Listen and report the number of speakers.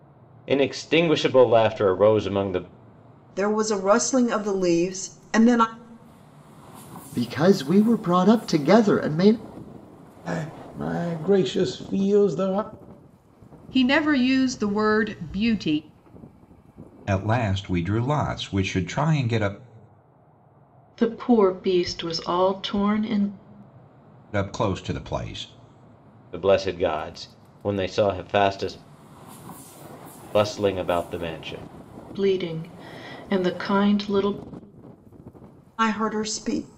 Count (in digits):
7